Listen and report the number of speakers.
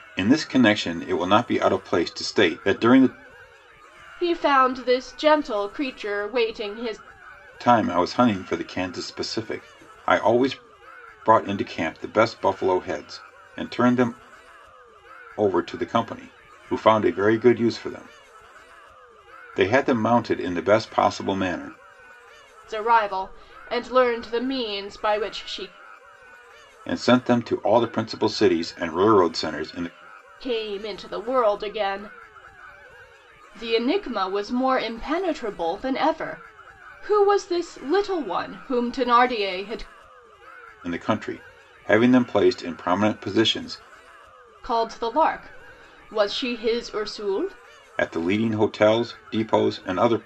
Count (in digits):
2